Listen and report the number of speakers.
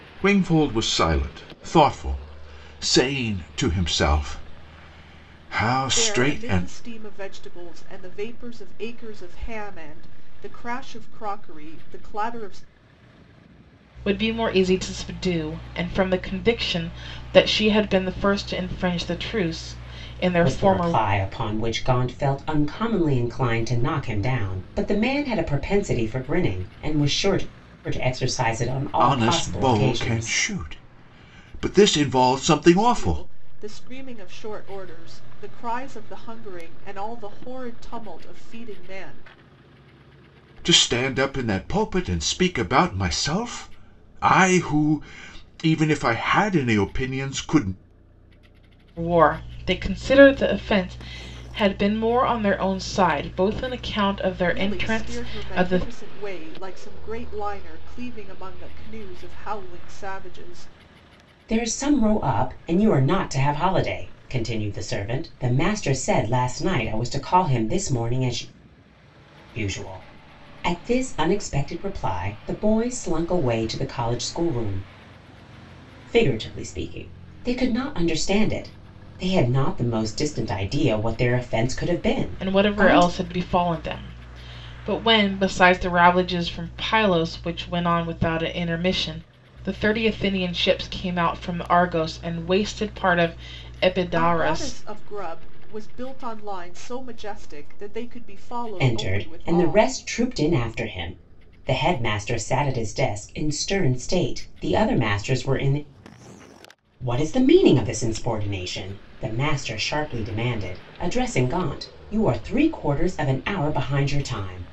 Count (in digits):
4